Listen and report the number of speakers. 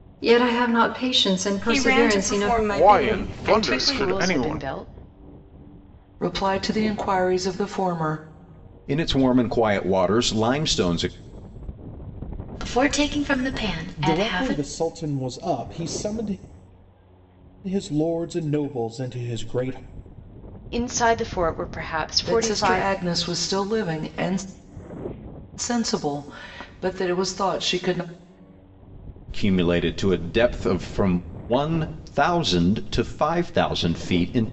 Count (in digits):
8